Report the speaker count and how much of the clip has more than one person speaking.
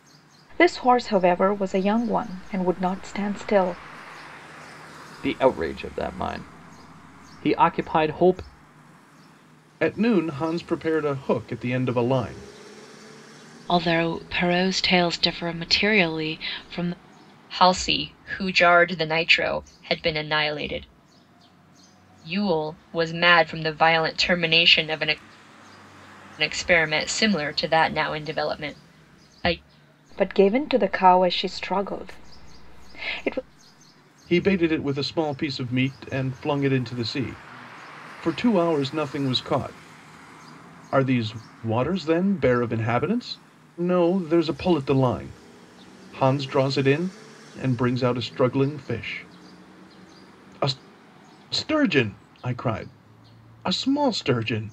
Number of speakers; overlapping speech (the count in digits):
5, no overlap